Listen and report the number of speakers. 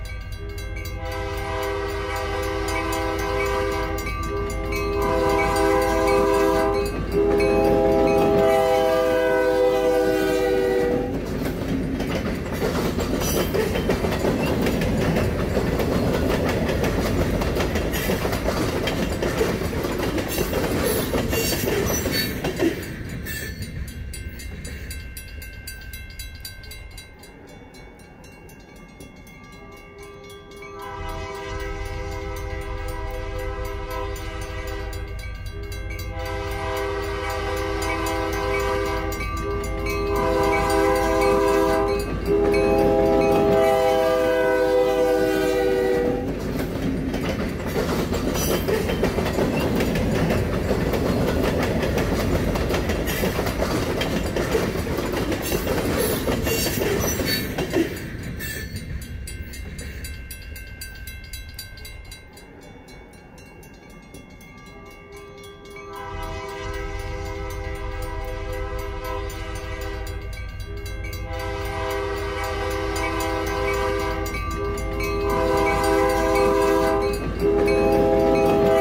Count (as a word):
zero